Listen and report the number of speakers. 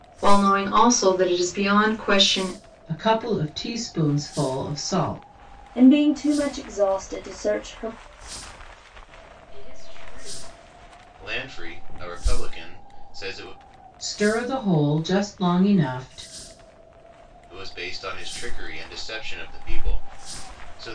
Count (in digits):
5